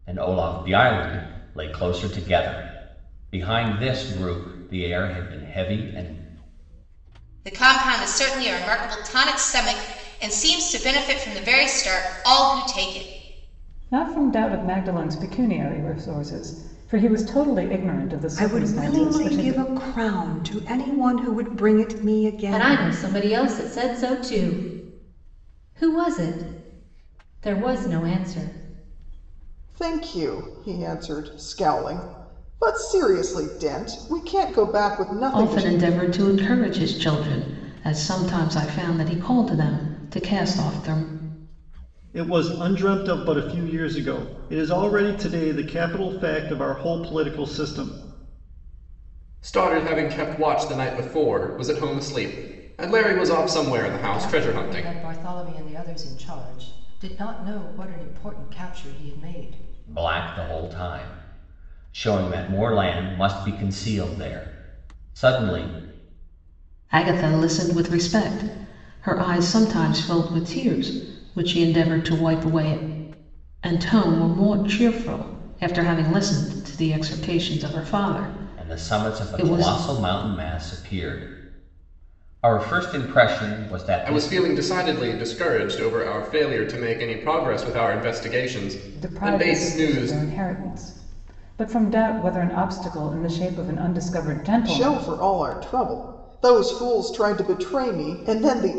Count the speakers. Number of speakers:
10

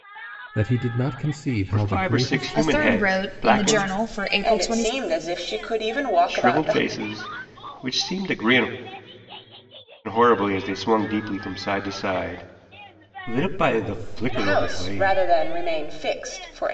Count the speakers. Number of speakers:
4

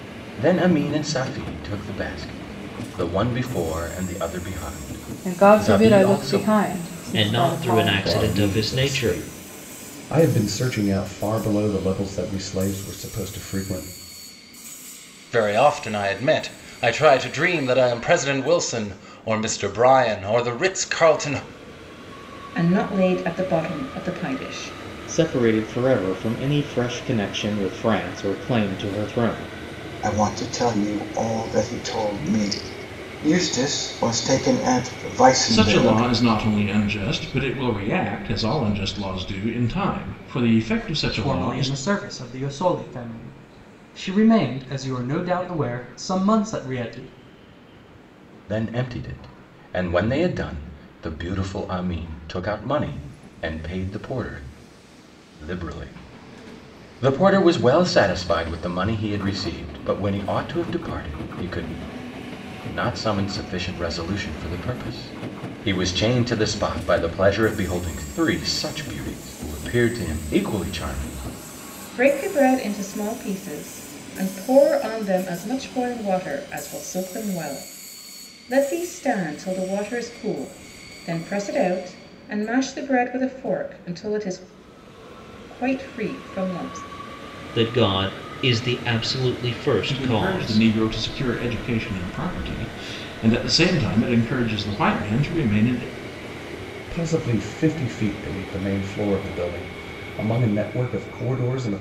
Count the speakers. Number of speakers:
10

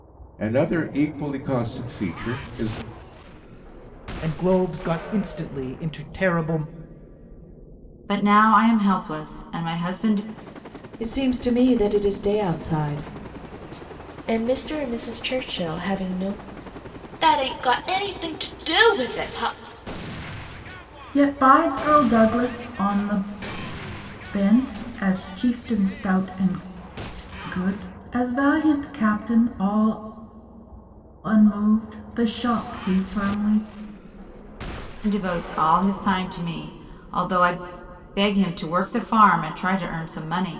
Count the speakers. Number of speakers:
7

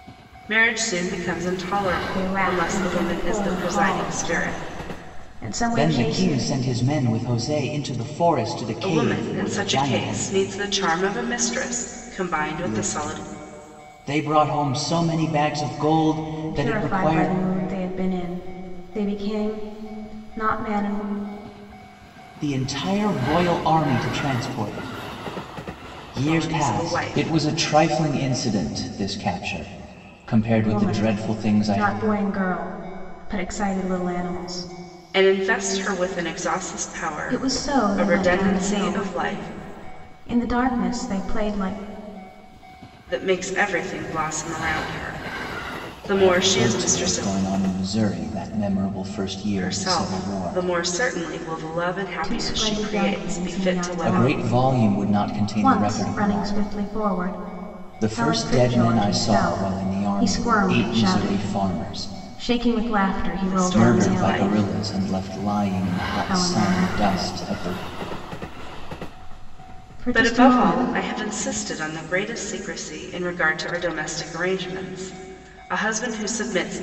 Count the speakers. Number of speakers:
3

